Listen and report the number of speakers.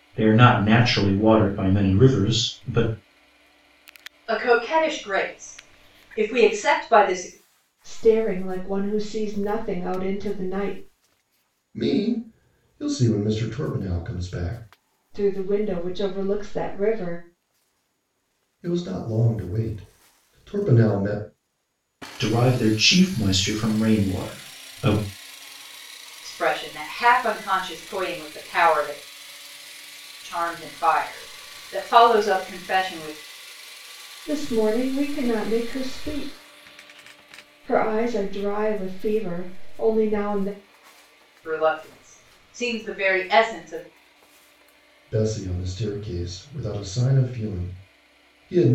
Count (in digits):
4